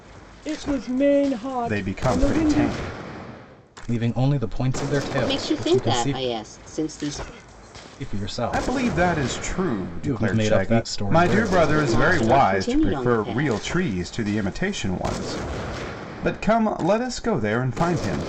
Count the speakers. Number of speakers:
four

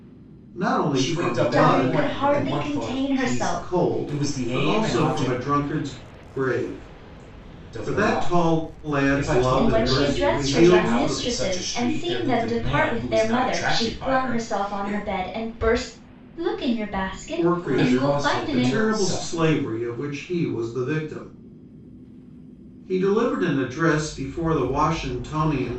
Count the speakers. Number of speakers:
three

